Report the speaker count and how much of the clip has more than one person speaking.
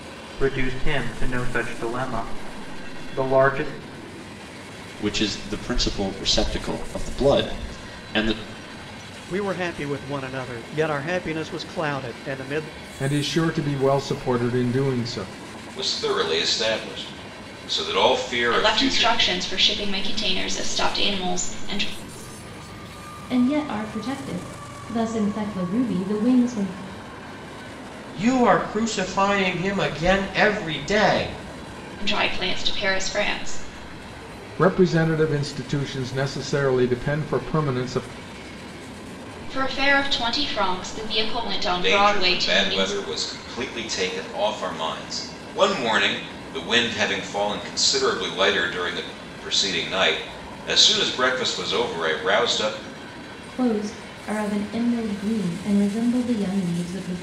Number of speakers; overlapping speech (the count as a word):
eight, about 3%